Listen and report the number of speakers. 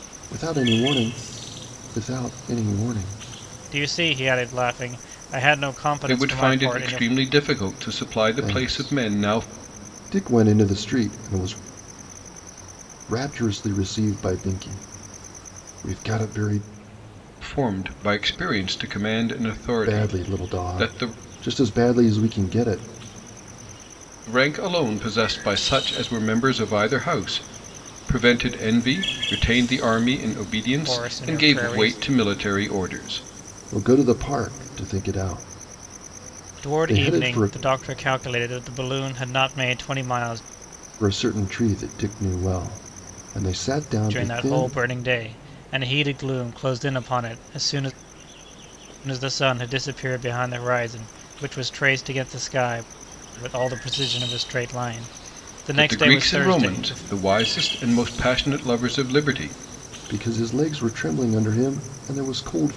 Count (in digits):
3